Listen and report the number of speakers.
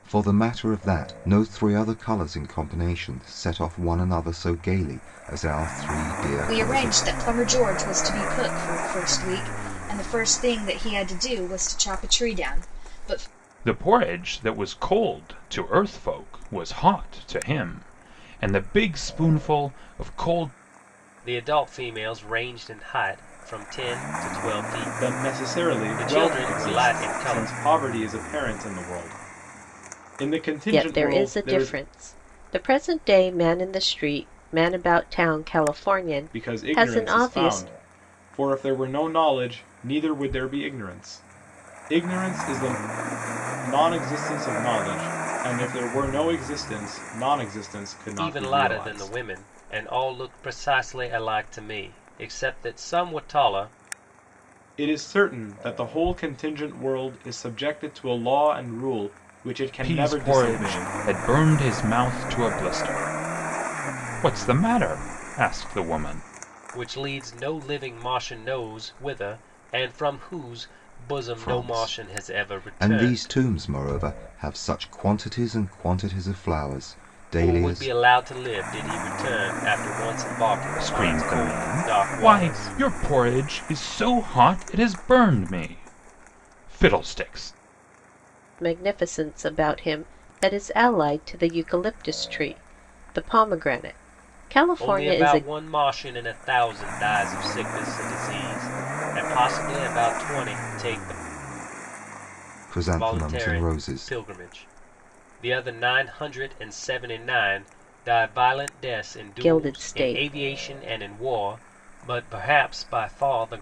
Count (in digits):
6